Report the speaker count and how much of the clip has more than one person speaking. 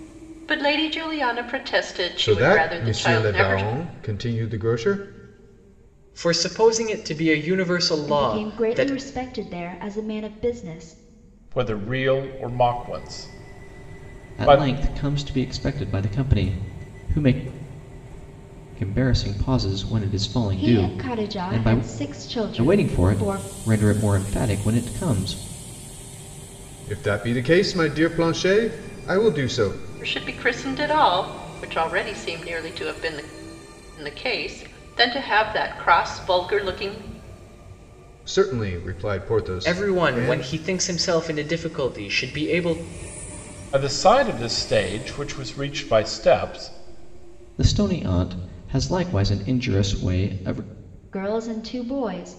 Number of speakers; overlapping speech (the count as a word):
six, about 11%